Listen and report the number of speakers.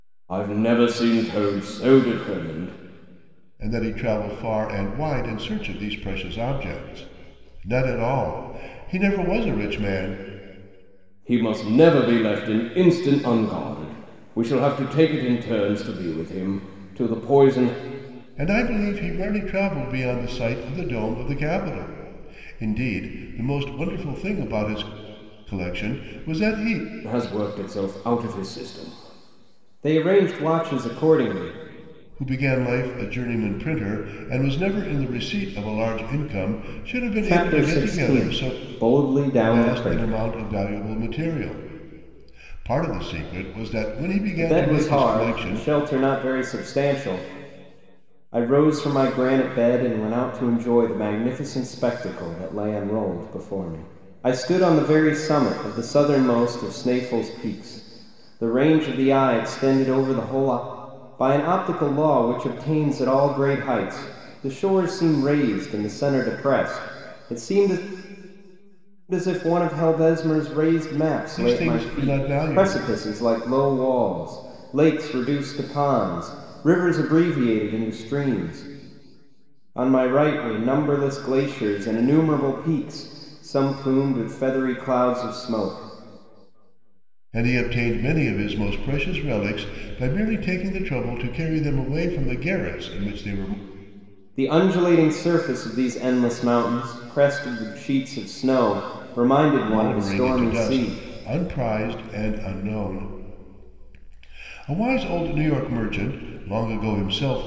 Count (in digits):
2